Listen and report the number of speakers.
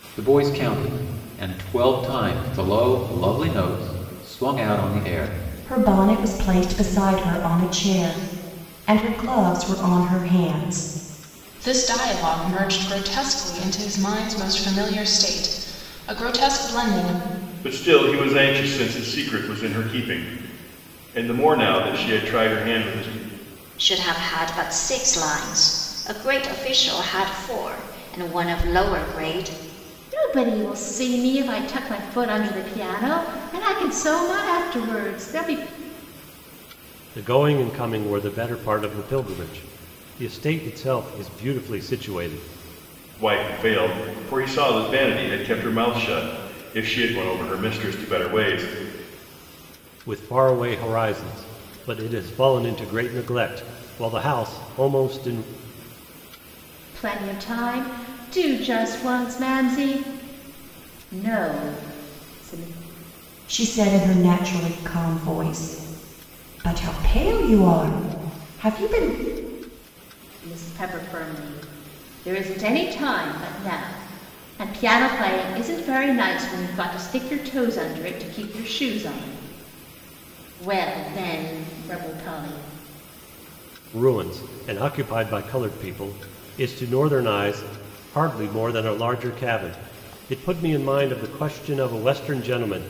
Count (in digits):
7